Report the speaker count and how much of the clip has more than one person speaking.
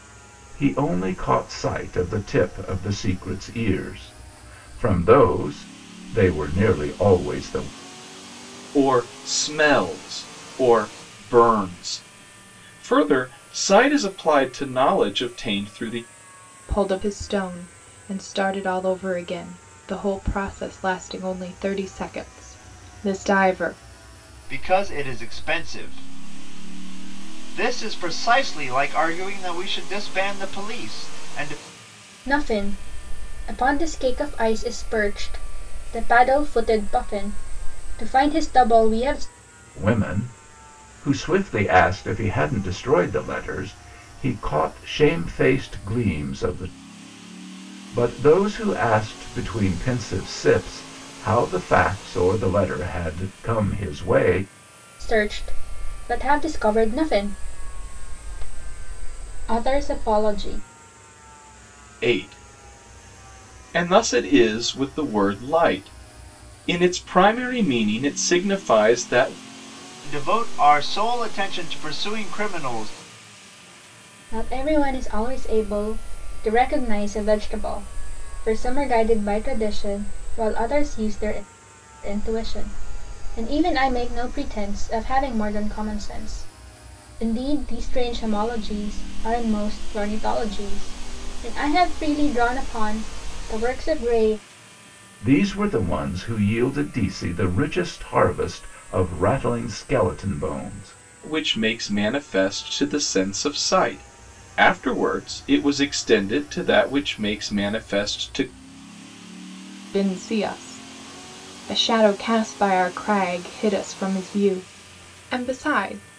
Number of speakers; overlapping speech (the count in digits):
5, no overlap